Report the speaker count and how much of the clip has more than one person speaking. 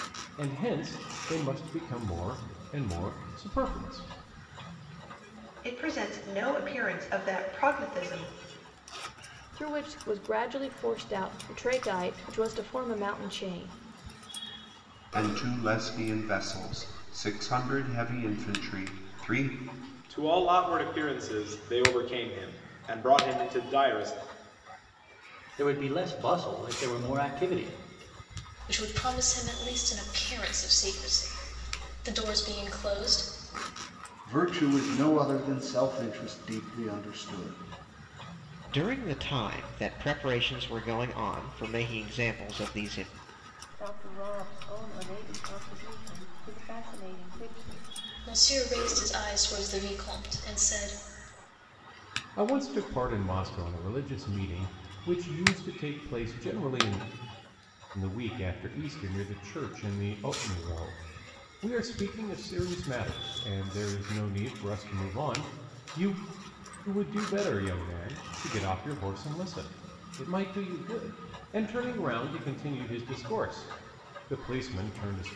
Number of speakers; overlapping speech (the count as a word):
ten, no overlap